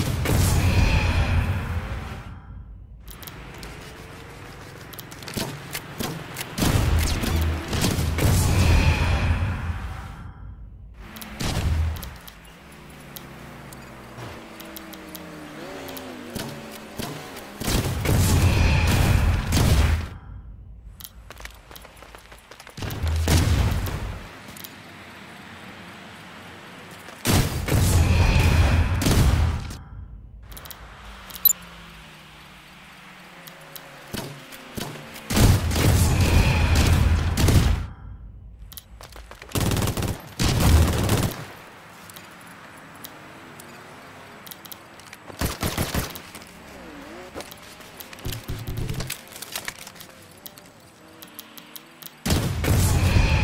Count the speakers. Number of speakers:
0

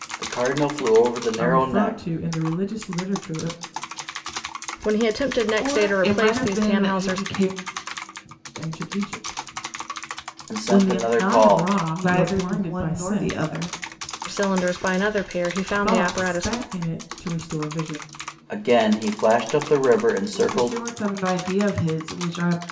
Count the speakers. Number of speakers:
4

